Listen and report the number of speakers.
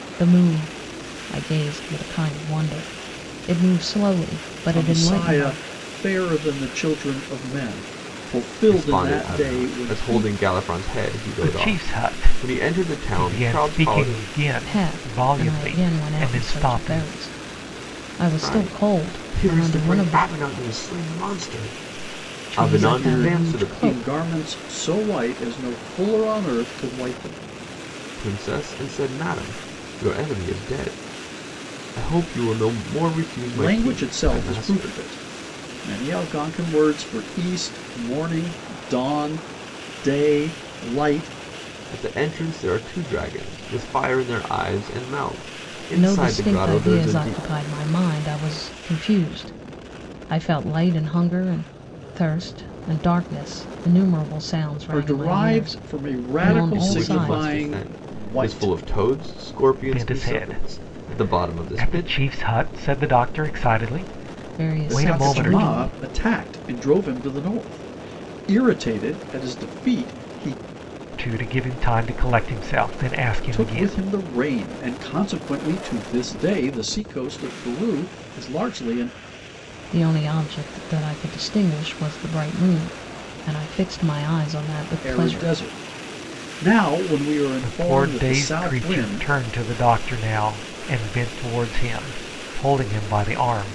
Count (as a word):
four